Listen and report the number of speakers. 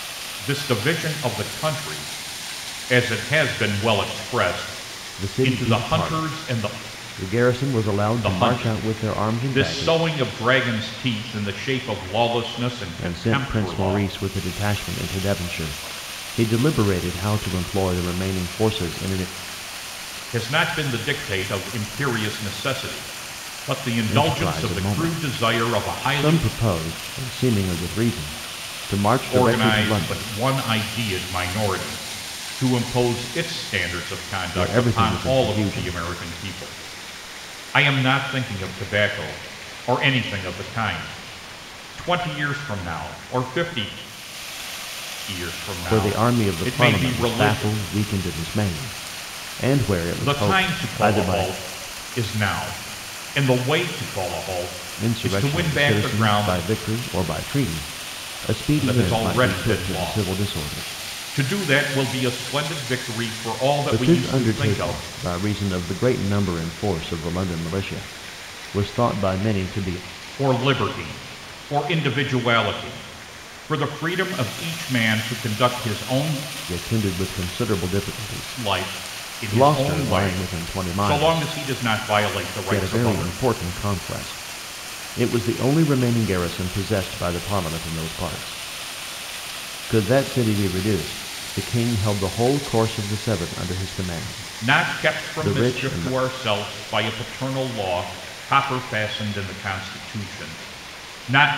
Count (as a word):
two